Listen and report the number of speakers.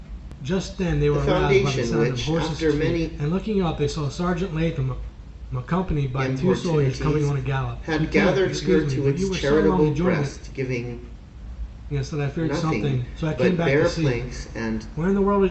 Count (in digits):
2